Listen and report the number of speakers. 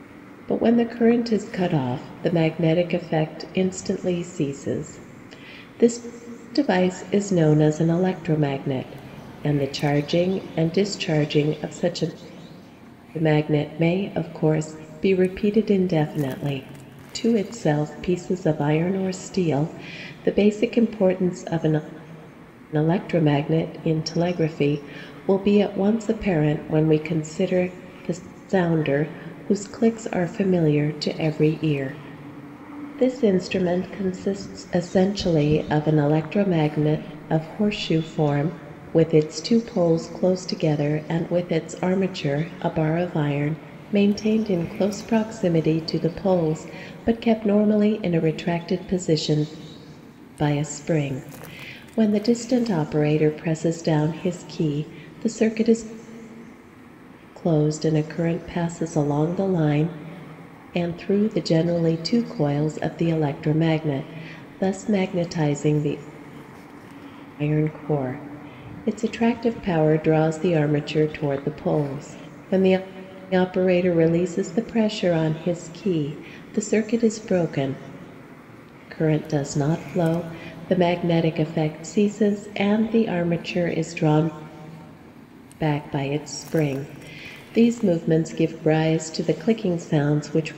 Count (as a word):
one